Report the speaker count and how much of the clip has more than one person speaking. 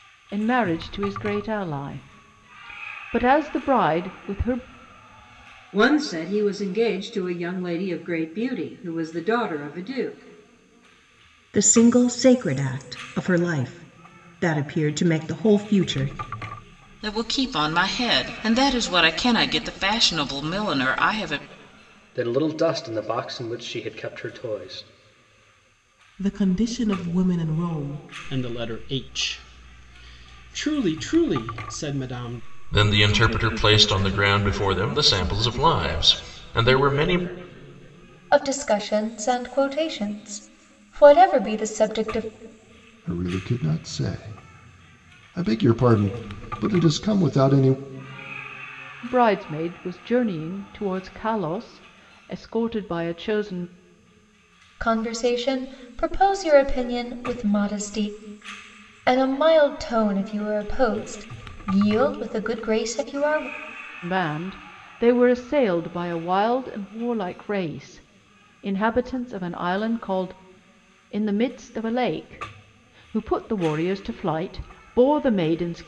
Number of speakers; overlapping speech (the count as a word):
ten, no overlap